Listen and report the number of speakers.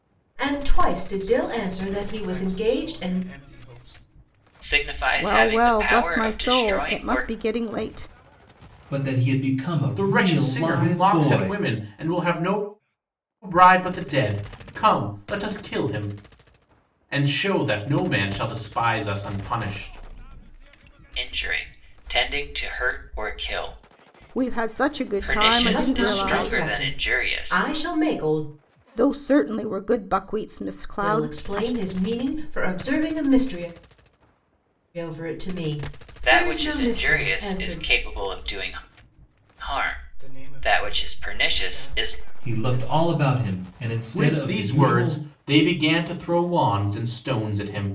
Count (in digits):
6